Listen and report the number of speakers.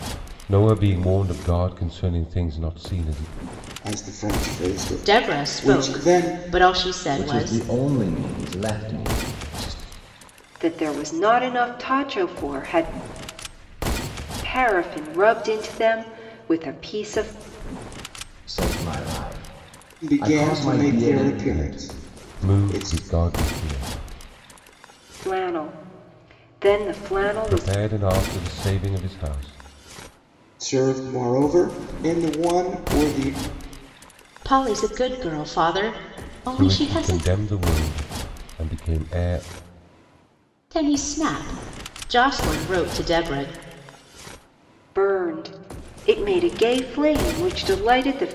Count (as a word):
five